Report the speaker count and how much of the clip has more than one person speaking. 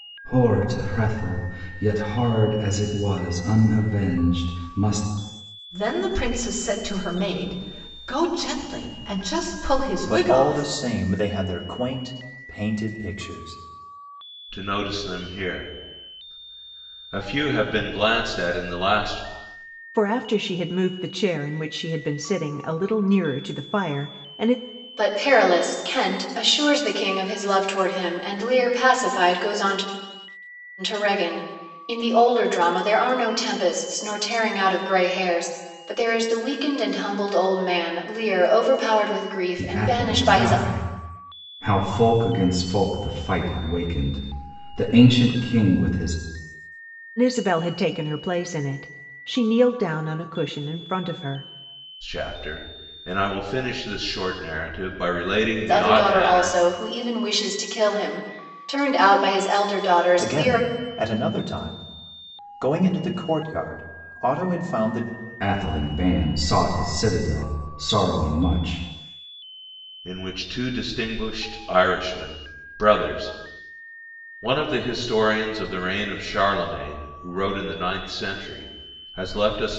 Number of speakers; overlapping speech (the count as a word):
six, about 4%